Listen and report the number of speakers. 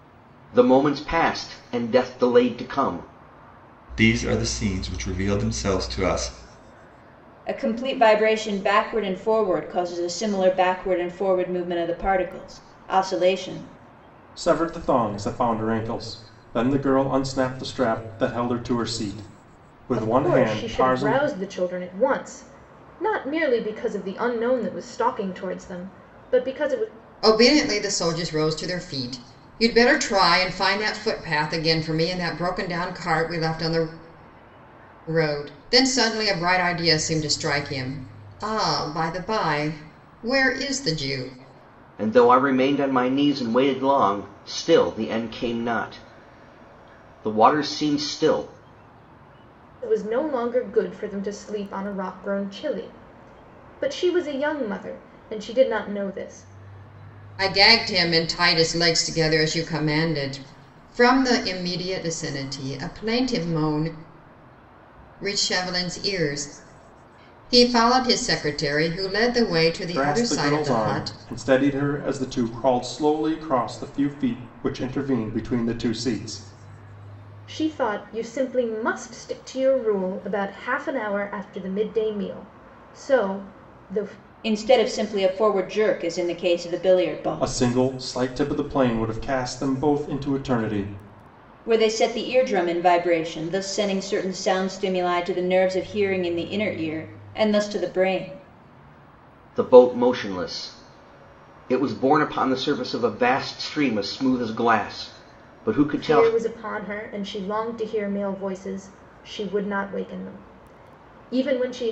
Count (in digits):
6